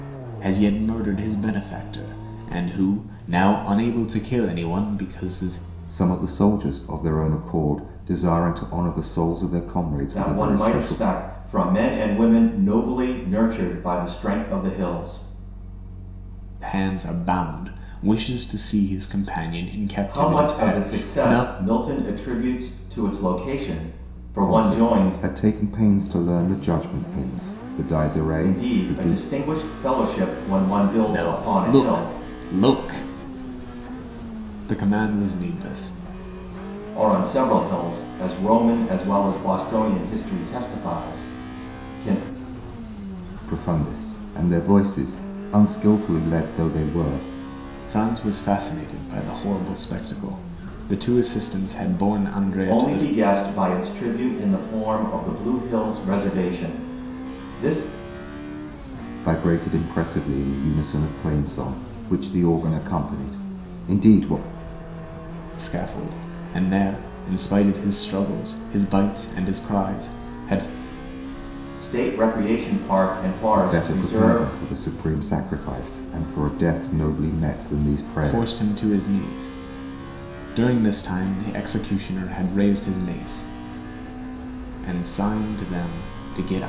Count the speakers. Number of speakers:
three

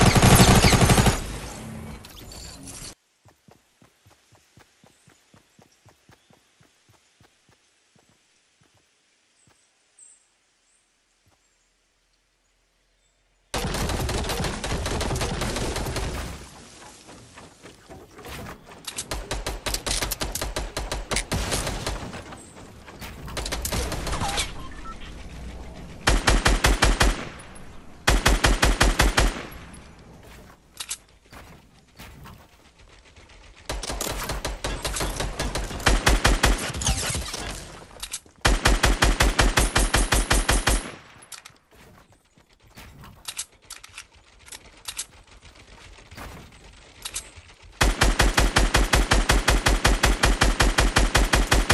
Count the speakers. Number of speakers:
zero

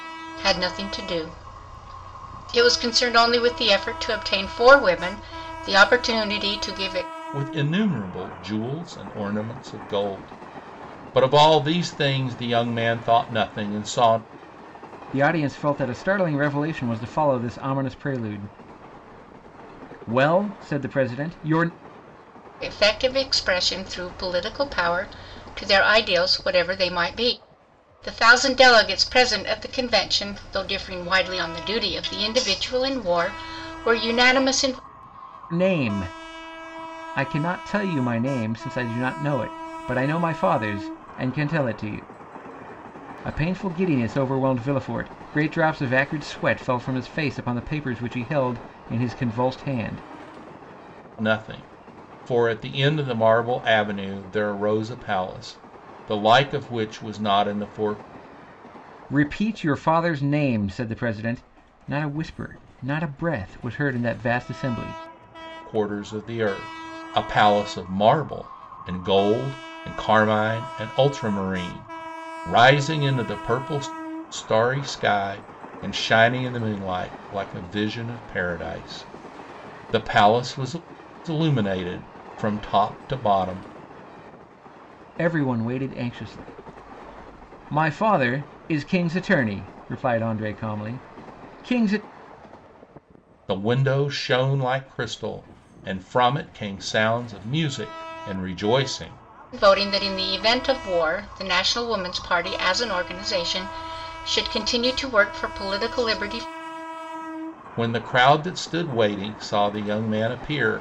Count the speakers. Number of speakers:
three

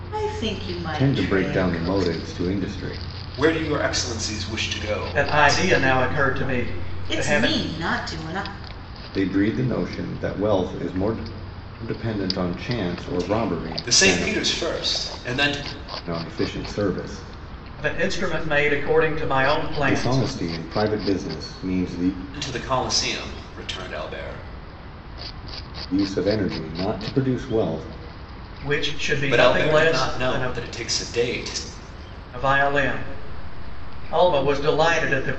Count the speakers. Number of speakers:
four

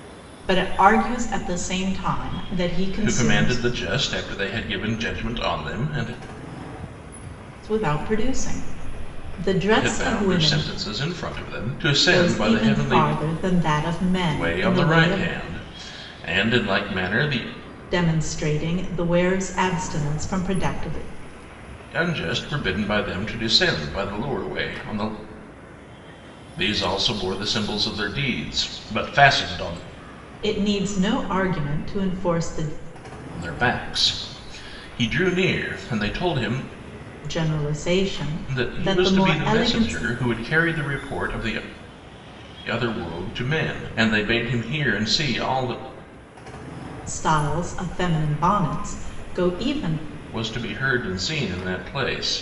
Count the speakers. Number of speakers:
two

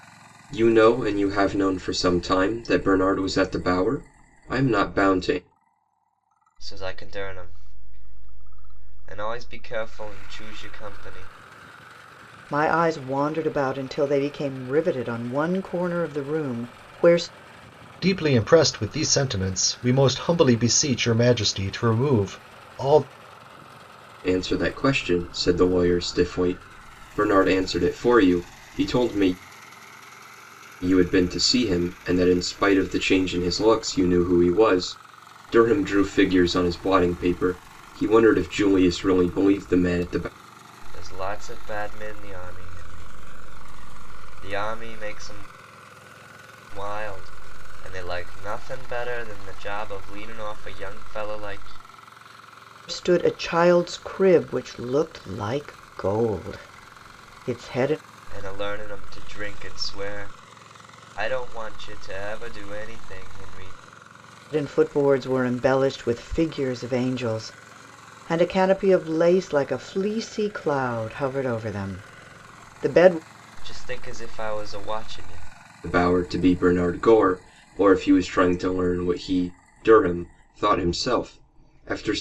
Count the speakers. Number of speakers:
four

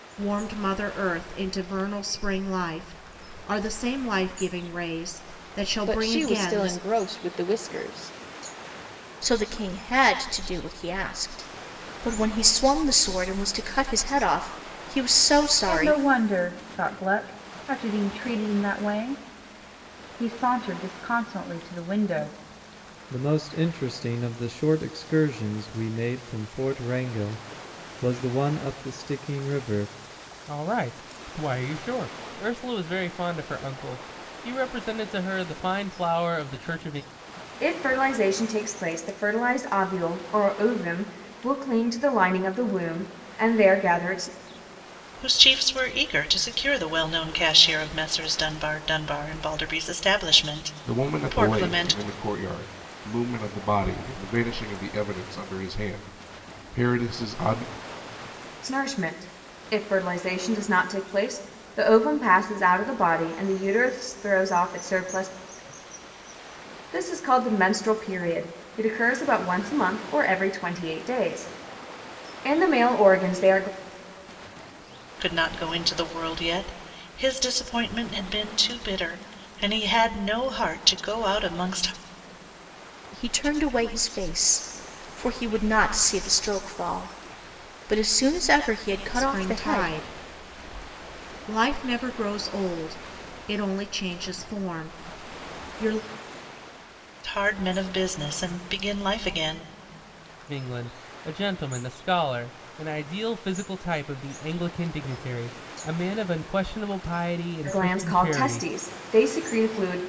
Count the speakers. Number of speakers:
nine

